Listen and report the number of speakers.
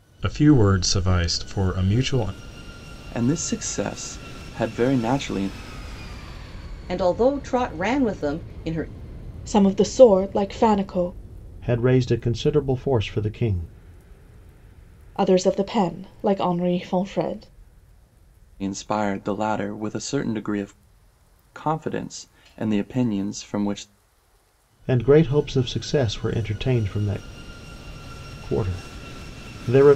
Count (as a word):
five